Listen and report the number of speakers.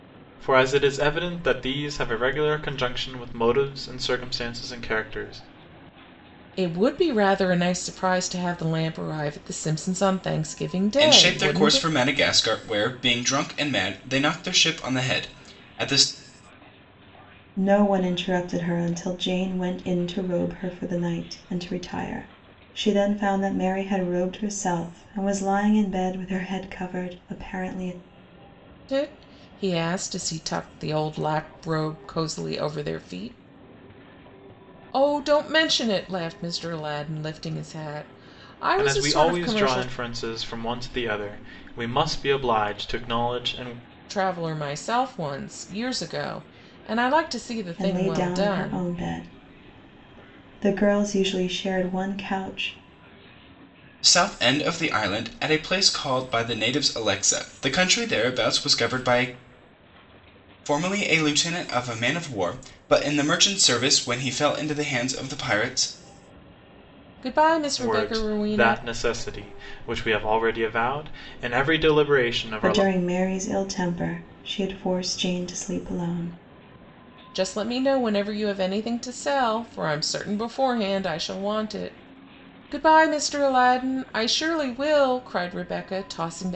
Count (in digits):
4